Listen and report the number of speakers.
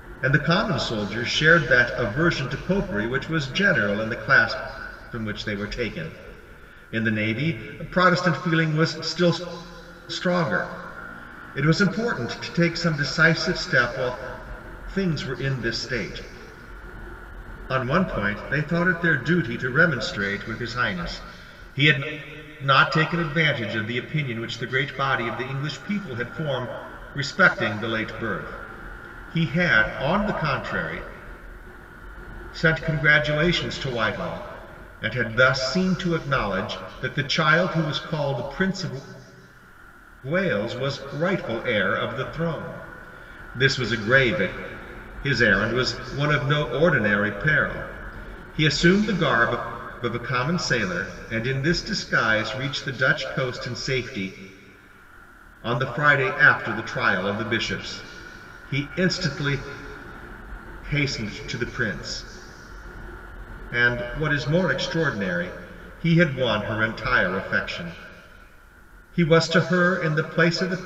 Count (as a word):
one